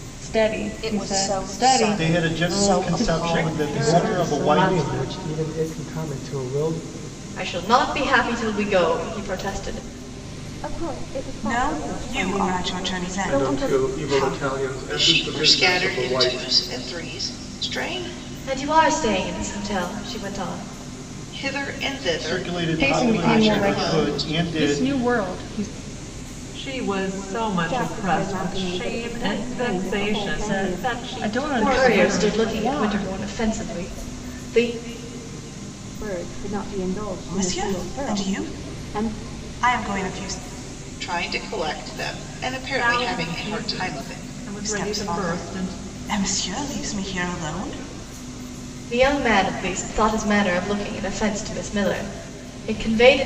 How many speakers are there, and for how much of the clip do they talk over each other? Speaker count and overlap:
ten, about 41%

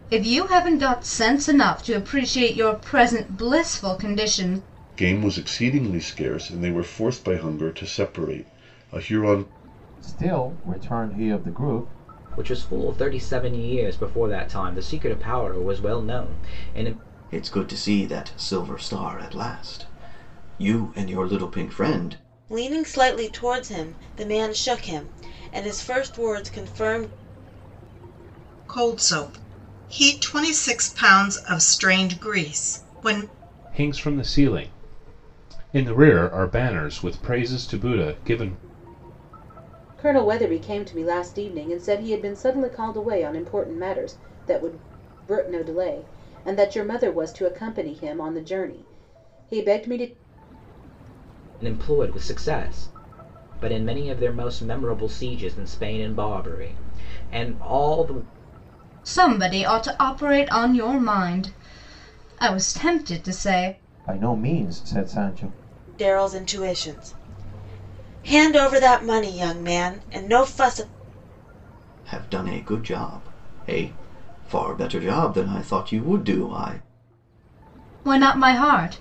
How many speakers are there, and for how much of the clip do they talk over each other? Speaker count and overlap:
nine, no overlap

